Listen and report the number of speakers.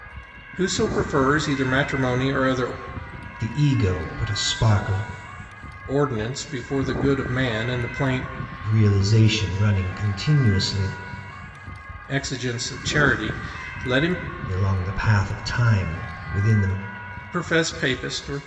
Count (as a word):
two